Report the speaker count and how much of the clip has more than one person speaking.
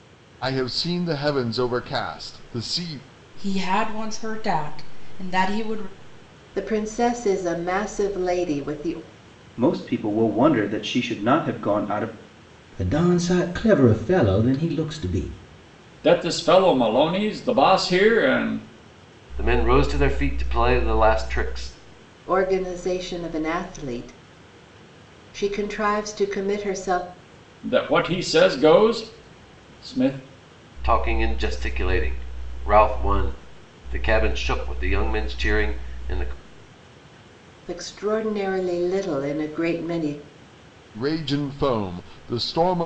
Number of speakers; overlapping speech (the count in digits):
7, no overlap